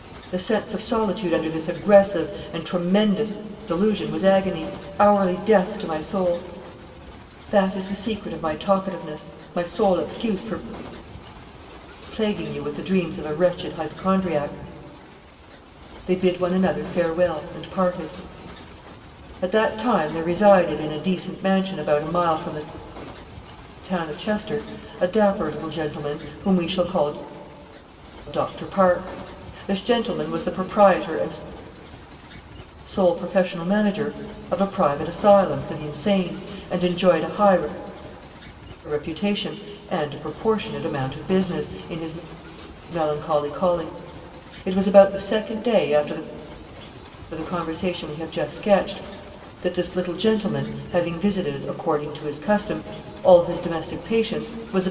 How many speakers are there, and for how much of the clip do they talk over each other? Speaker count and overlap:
one, no overlap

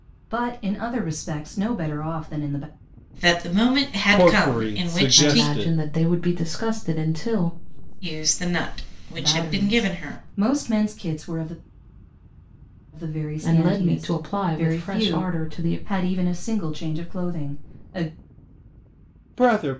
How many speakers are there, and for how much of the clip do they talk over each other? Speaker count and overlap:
five, about 48%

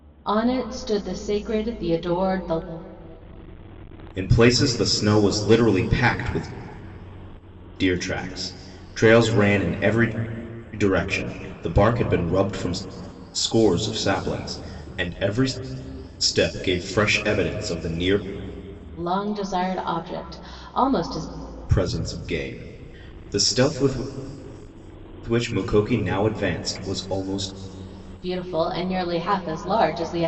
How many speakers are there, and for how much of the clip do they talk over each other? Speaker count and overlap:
two, no overlap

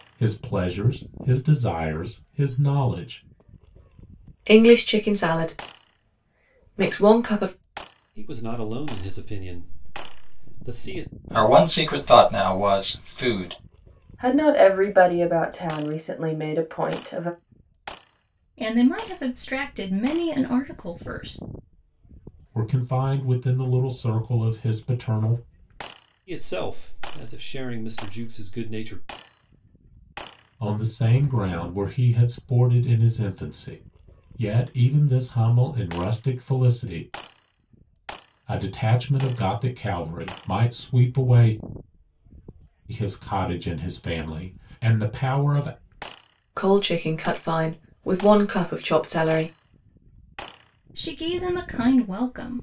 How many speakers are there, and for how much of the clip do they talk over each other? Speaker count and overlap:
six, no overlap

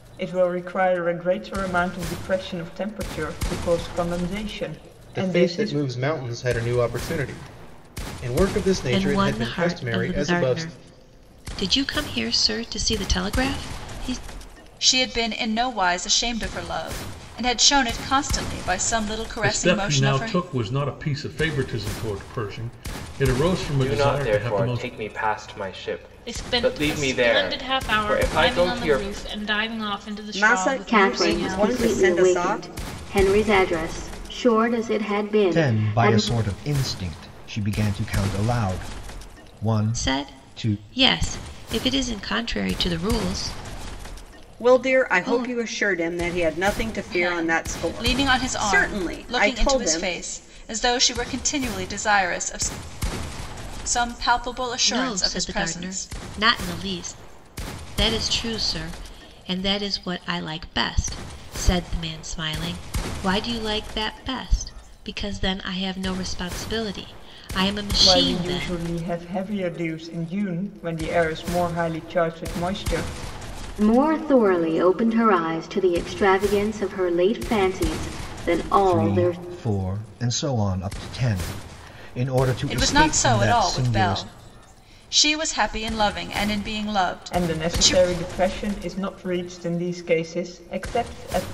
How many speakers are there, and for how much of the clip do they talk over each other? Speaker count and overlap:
ten, about 23%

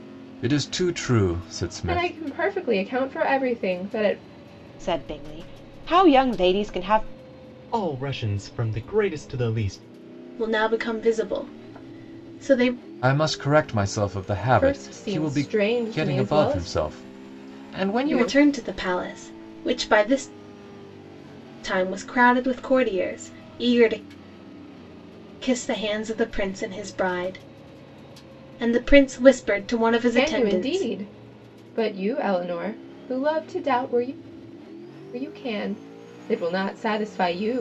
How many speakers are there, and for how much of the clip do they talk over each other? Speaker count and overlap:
five, about 9%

